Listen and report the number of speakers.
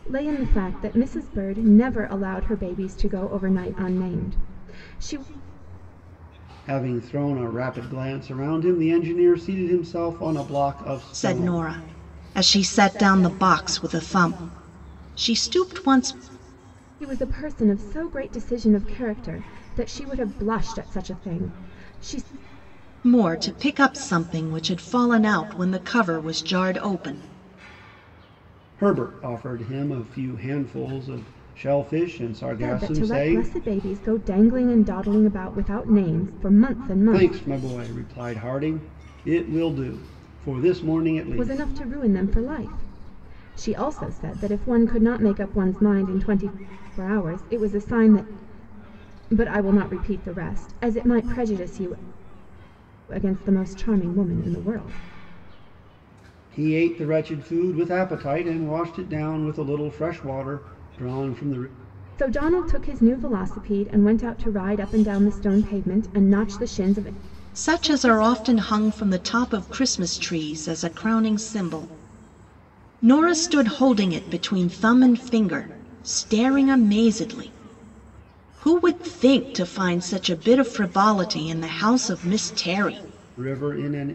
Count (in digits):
3